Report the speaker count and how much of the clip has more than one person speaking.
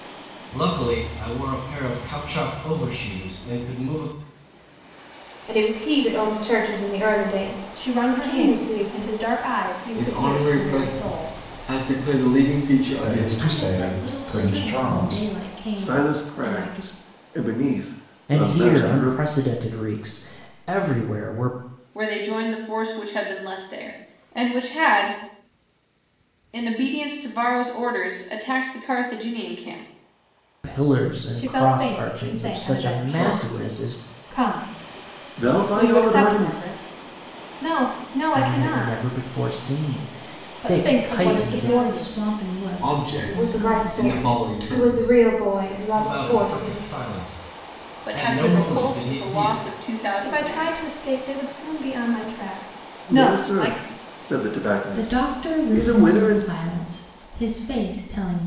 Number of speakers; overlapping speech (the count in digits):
9, about 36%